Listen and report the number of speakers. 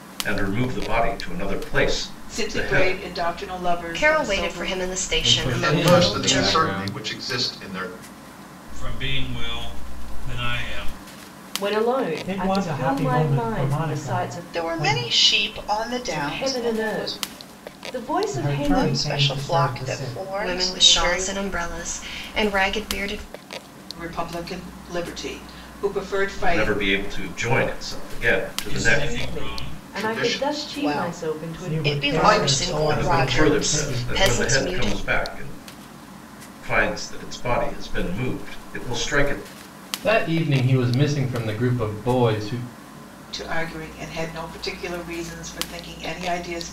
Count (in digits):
9